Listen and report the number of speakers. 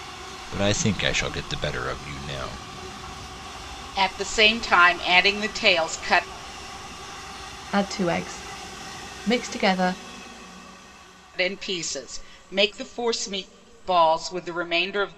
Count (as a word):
three